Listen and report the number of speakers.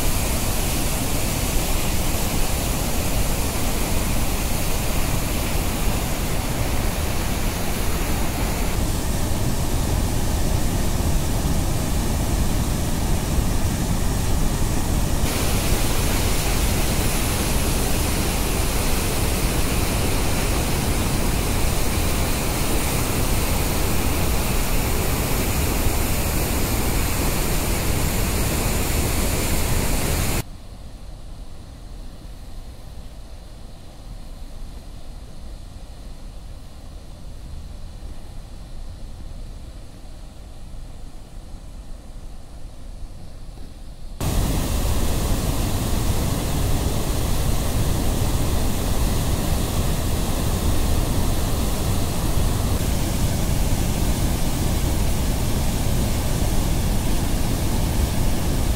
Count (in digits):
0